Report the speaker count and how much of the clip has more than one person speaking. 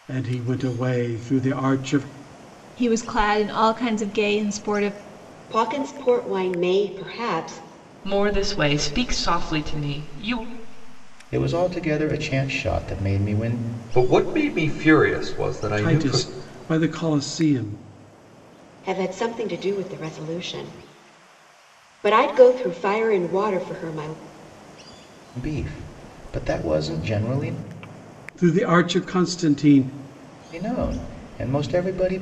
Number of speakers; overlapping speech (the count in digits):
6, about 2%